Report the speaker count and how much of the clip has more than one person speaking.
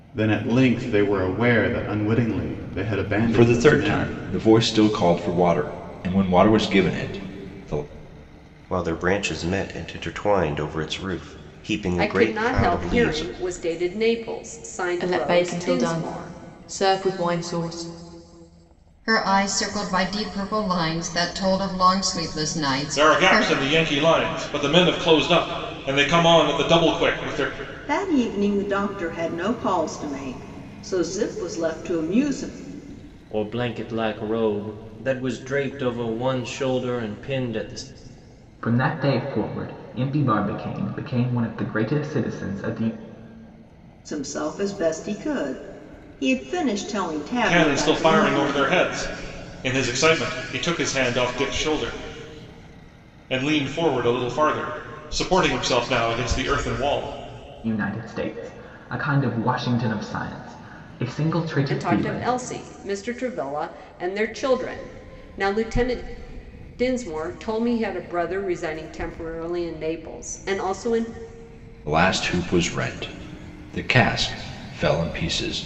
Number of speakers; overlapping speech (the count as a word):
ten, about 8%